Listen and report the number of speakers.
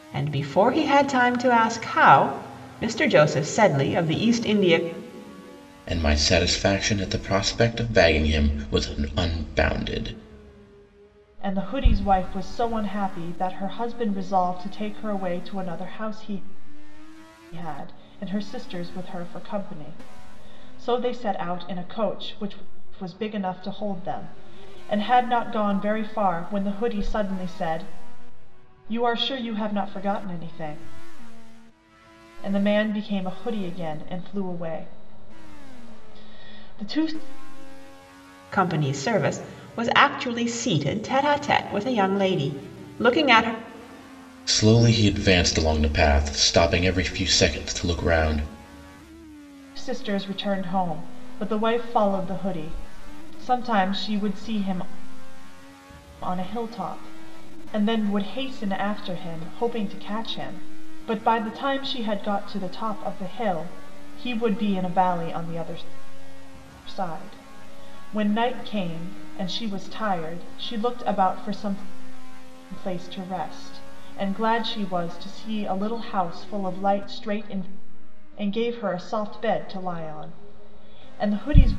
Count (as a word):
three